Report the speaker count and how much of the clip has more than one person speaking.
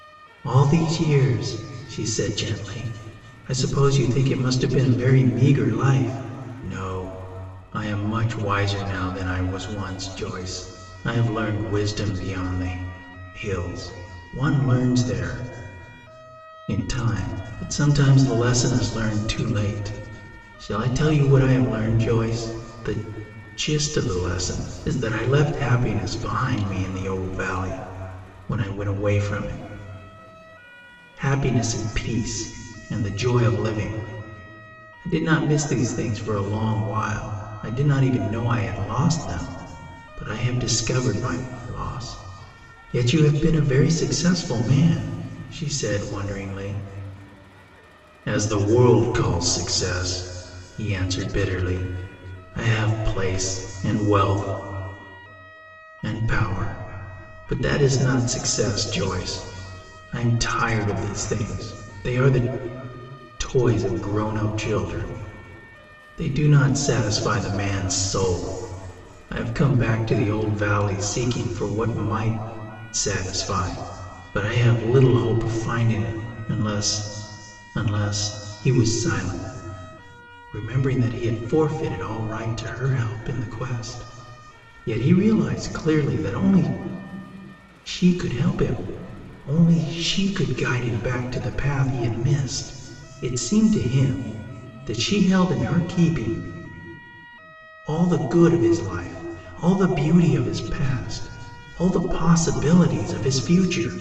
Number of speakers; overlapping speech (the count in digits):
1, no overlap